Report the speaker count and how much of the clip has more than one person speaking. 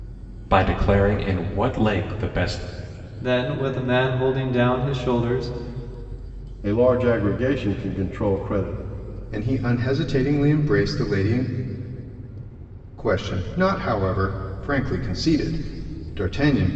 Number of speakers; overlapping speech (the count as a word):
four, no overlap